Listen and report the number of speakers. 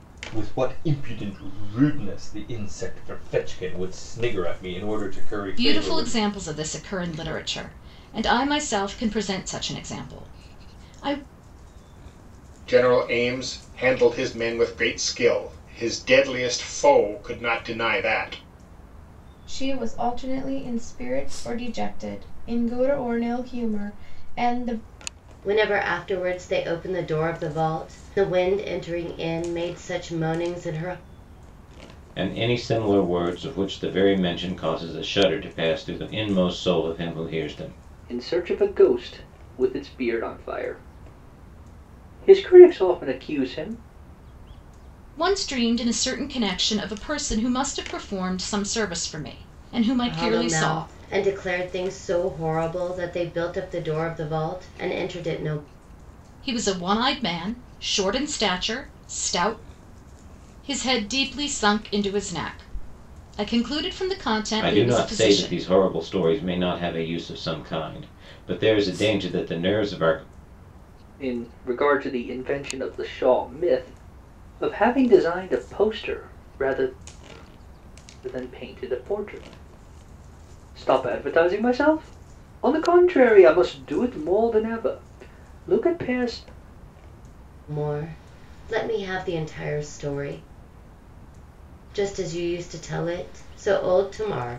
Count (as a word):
seven